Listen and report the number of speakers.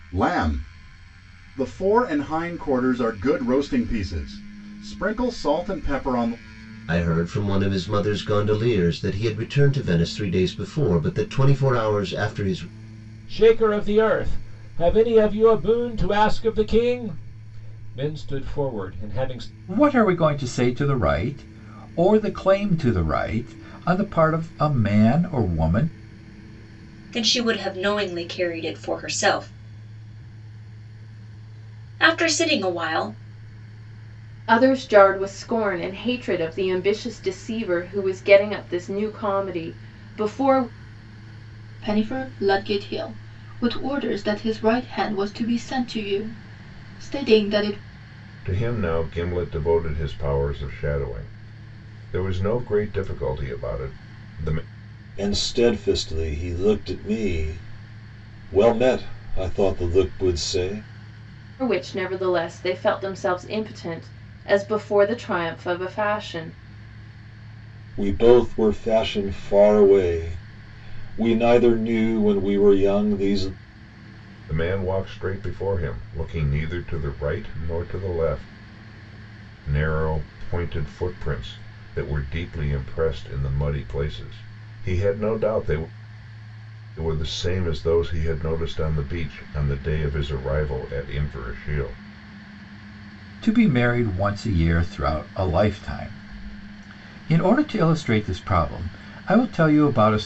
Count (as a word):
nine